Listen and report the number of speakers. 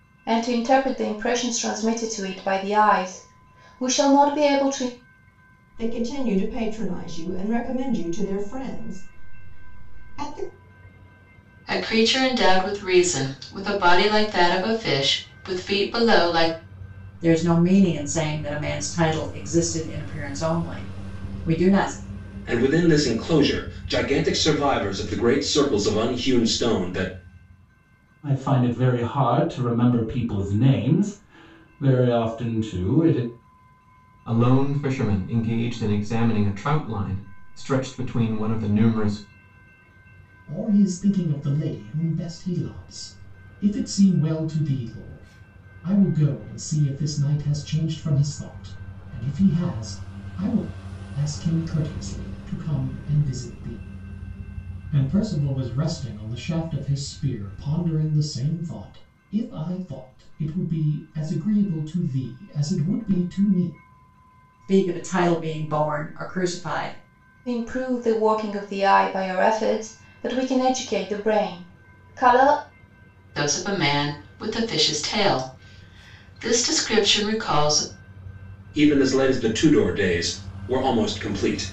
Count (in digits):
8